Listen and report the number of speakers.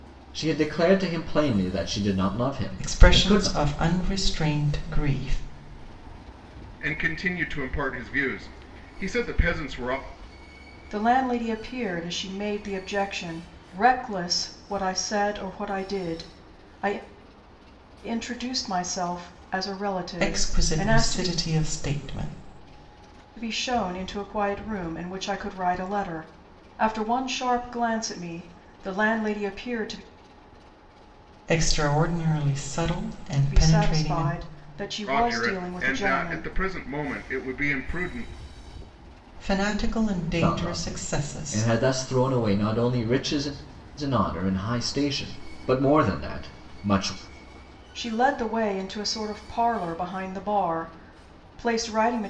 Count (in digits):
4